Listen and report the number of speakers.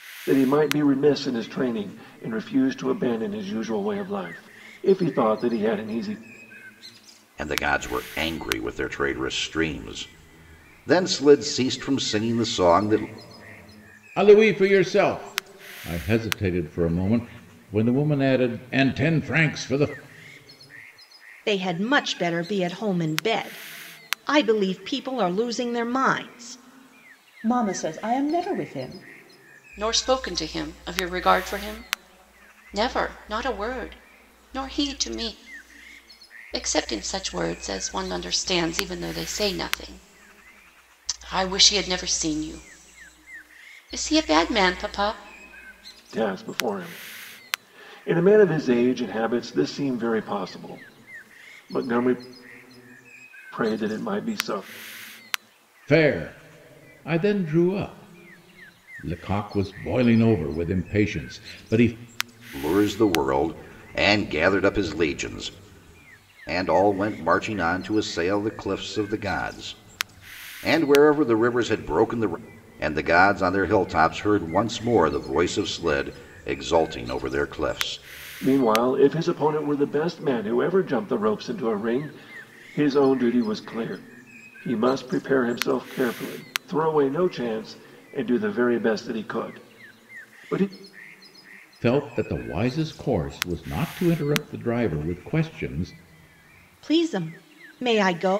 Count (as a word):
six